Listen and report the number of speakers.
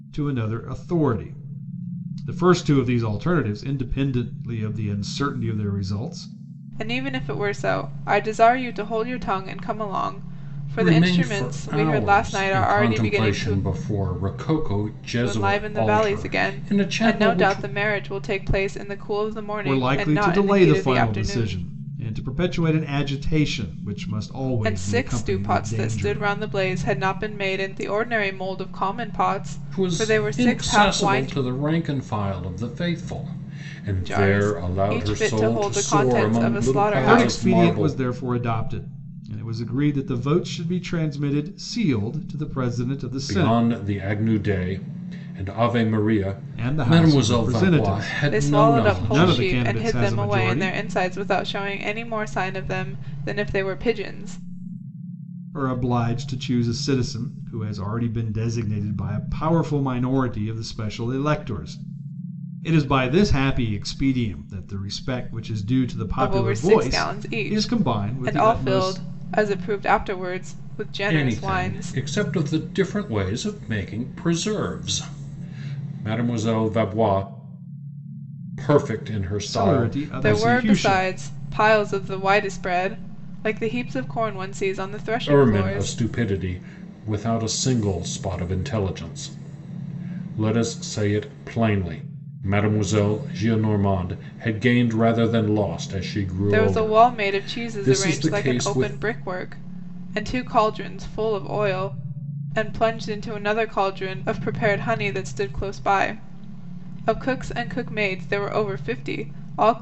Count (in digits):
3